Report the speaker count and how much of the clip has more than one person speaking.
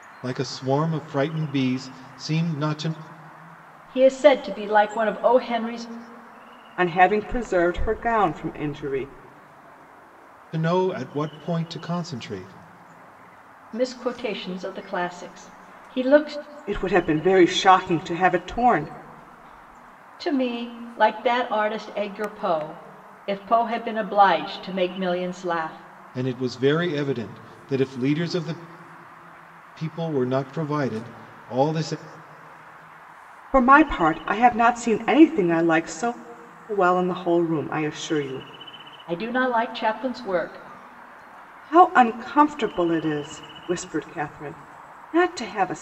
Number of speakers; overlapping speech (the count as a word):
three, no overlap